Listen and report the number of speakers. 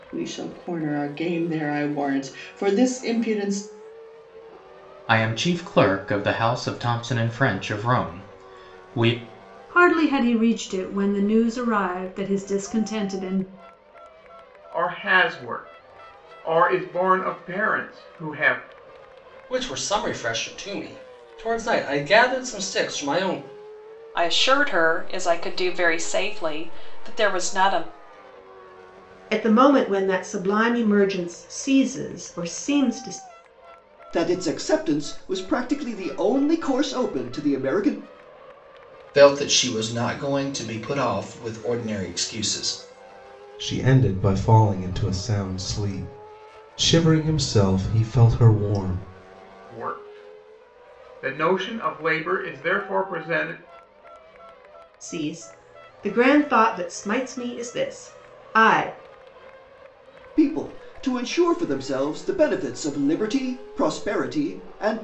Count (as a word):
ten